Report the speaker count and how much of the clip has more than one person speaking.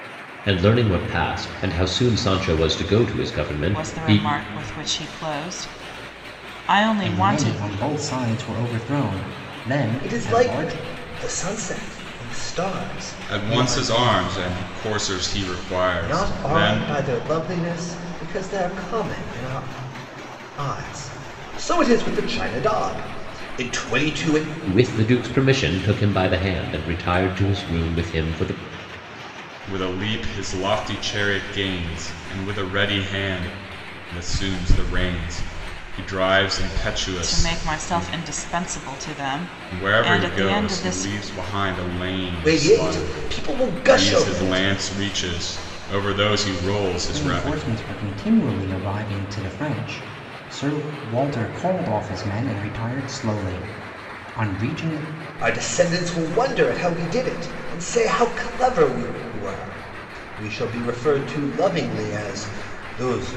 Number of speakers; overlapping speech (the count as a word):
five, about 13%